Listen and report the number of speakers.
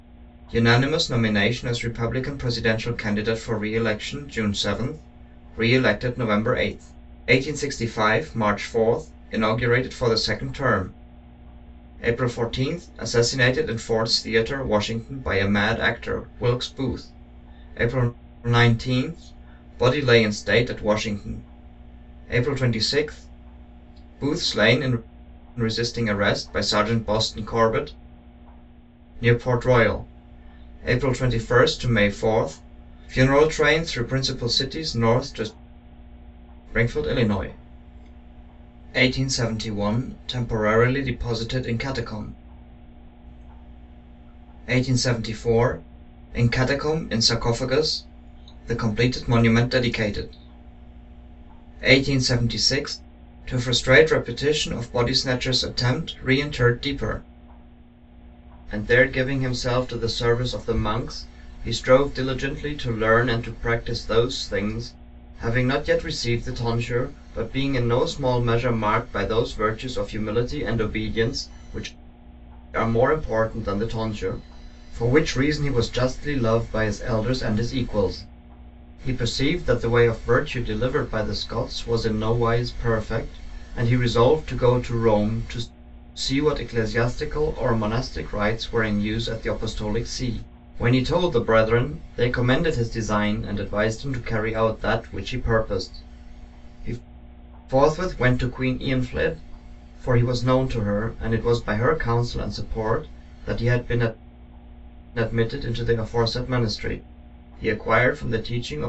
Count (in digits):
1